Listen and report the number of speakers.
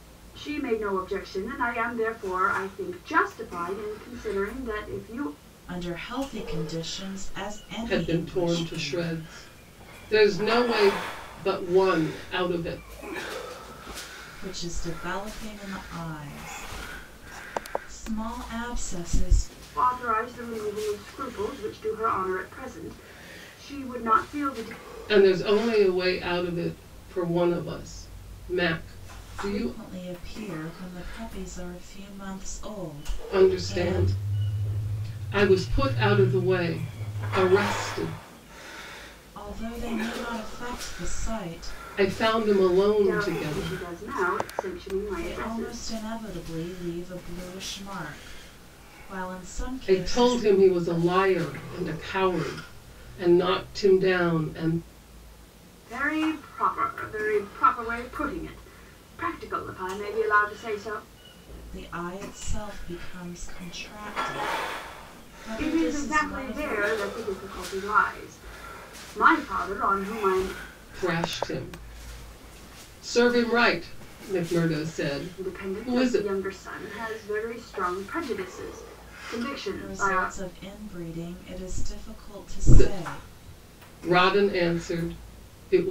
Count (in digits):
3